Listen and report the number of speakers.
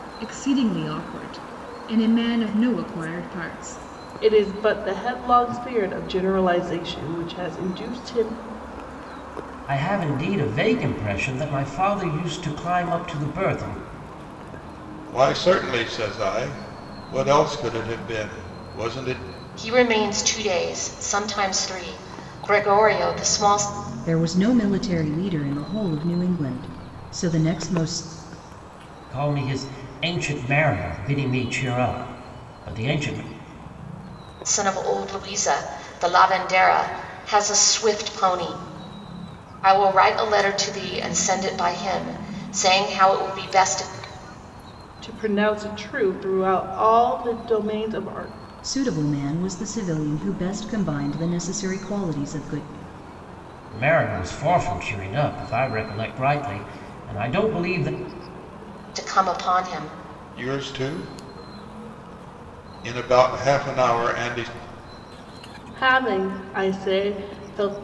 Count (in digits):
6